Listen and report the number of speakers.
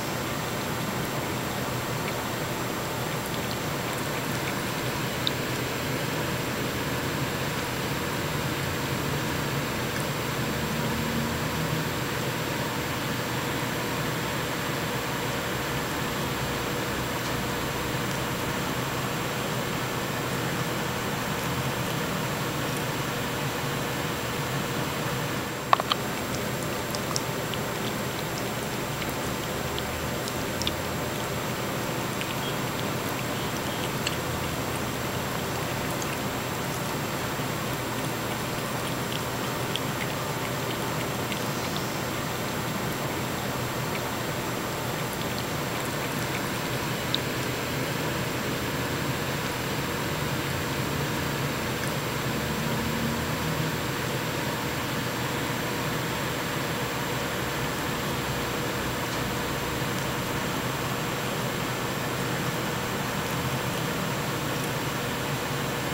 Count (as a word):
zero